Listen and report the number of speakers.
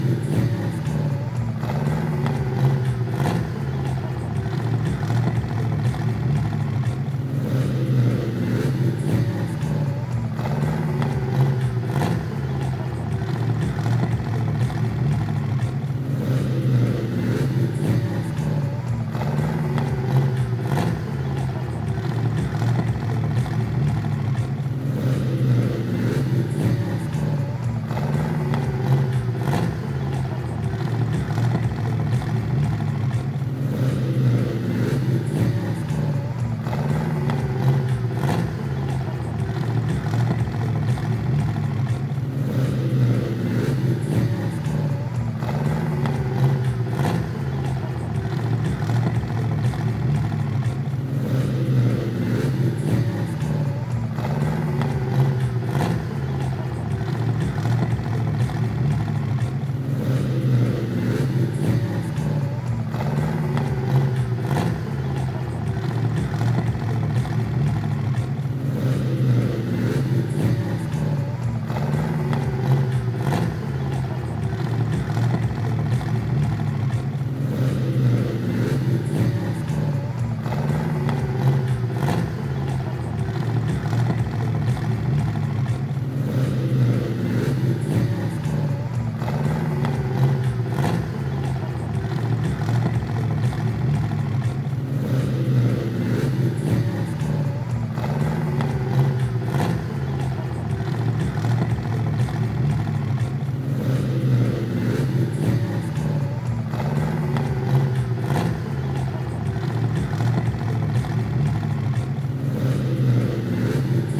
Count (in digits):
0